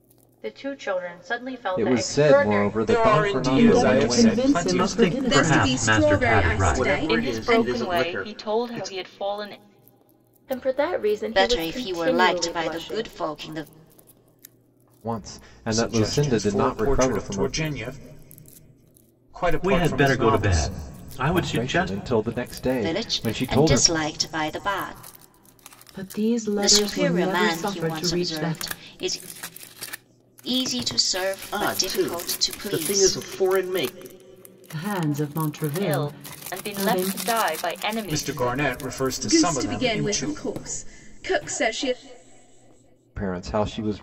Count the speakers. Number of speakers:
ten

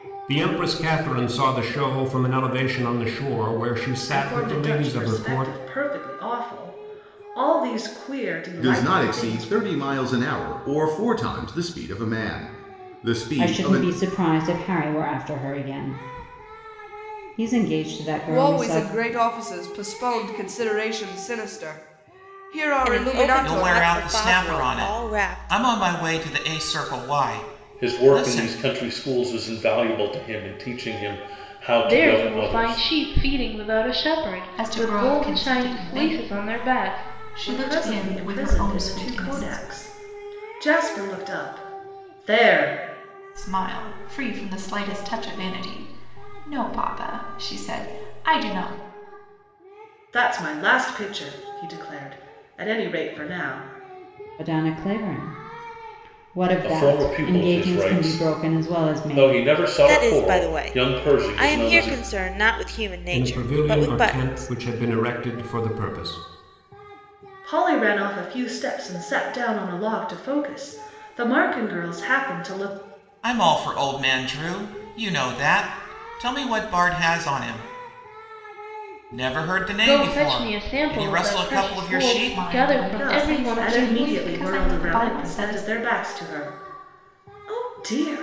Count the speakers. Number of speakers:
ten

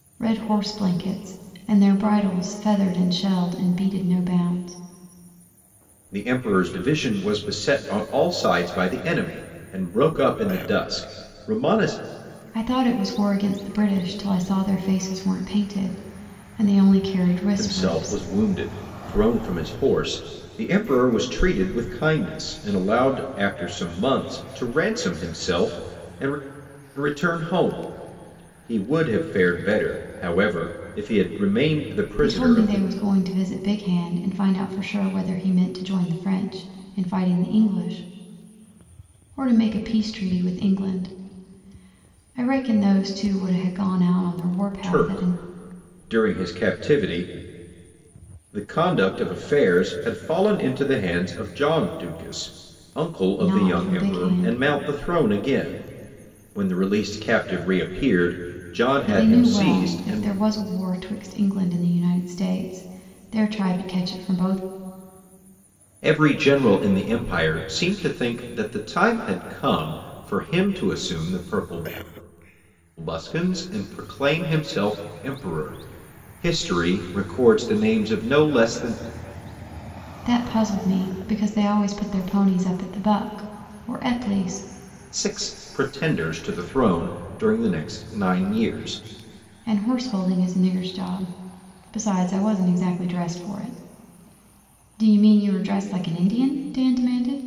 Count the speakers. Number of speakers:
two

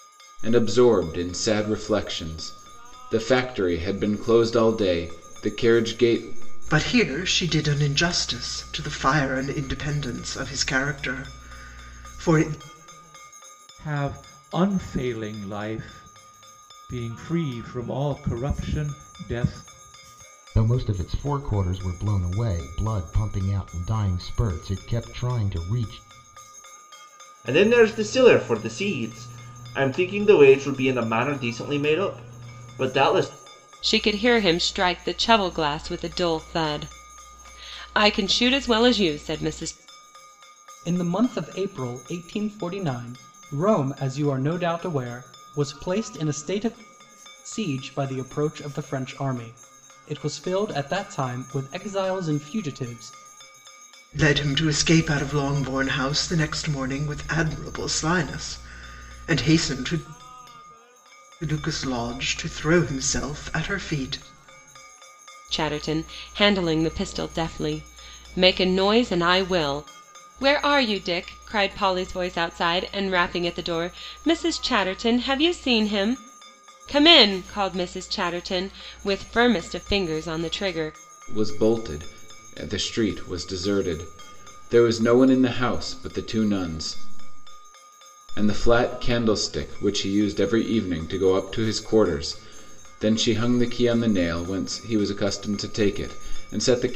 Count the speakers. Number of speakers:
seven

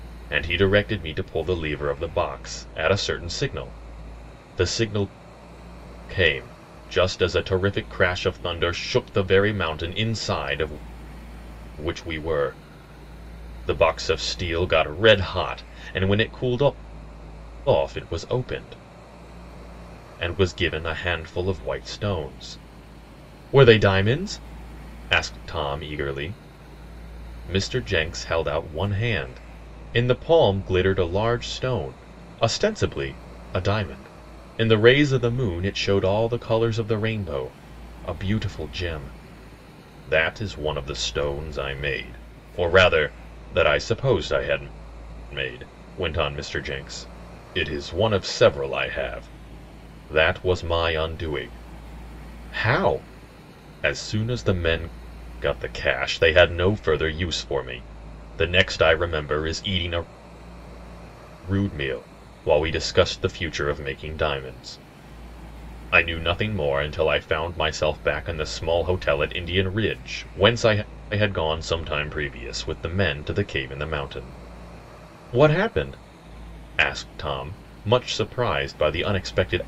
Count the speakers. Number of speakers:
one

